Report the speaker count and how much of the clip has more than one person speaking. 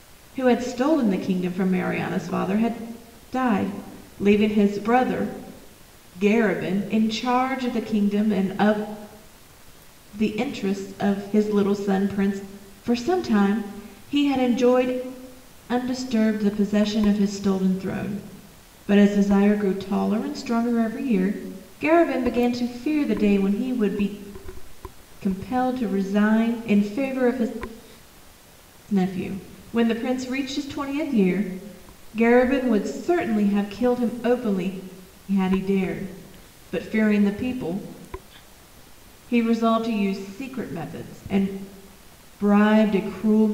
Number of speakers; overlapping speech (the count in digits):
1, no overlap